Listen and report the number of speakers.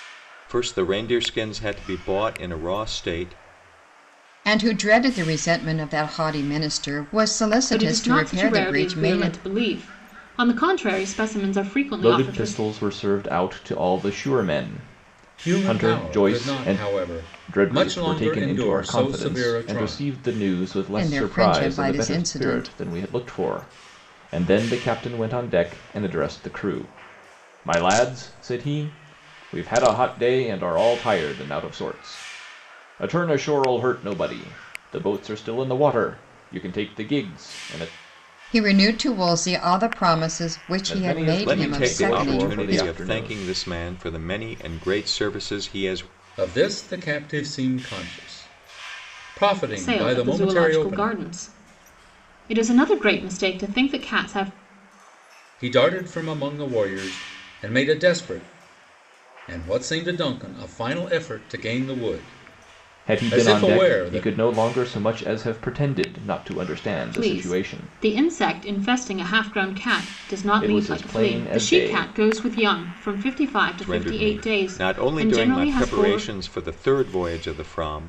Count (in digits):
5